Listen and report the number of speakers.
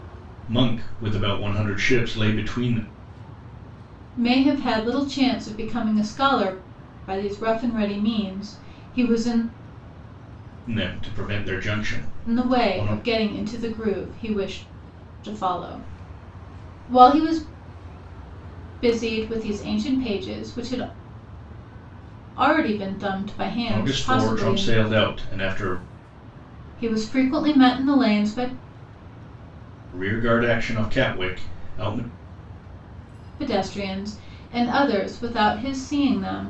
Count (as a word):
two